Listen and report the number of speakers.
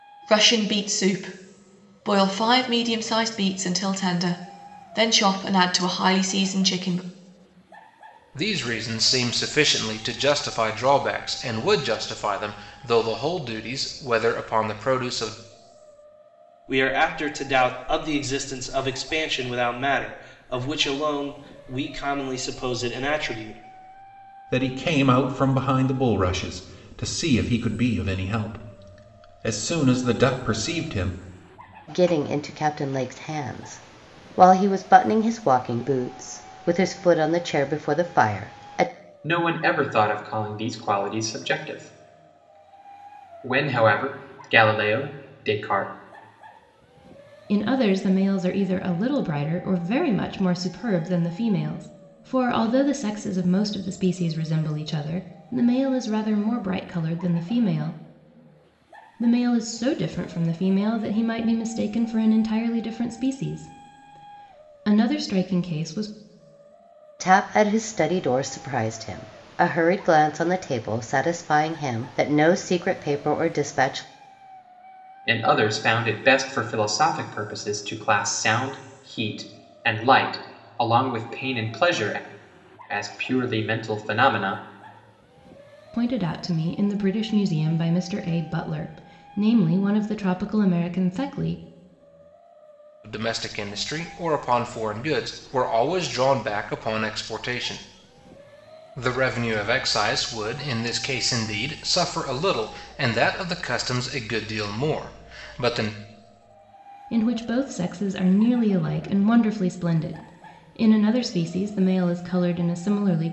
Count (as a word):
seven